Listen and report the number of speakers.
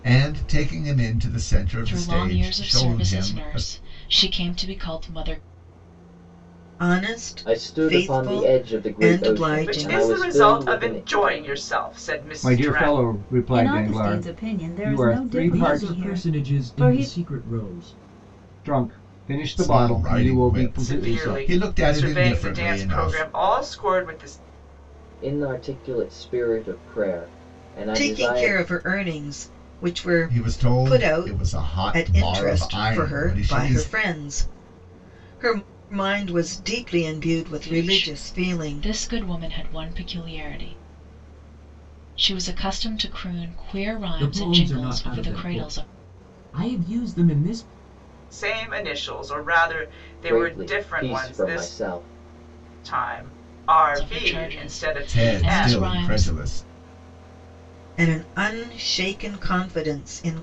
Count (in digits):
8